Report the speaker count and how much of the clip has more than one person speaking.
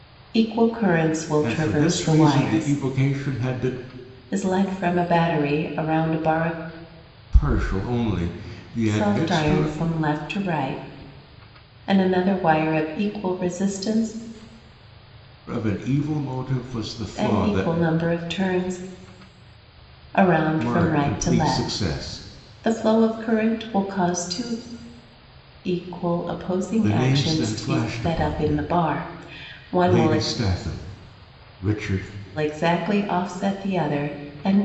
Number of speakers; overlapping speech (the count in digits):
2, about 18%